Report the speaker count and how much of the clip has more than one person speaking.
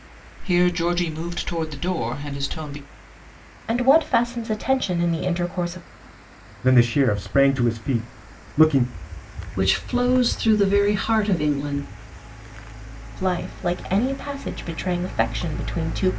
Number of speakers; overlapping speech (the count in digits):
4, no overlap